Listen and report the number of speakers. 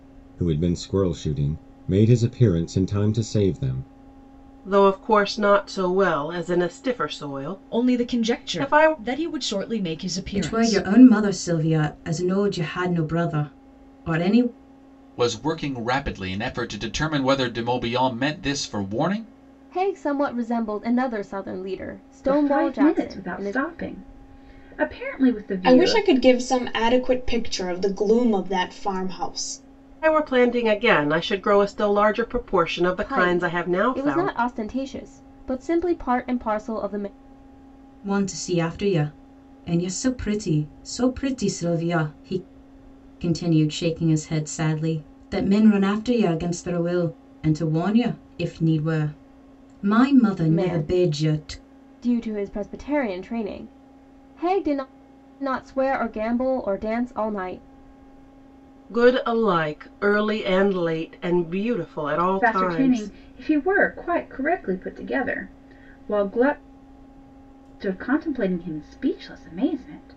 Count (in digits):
8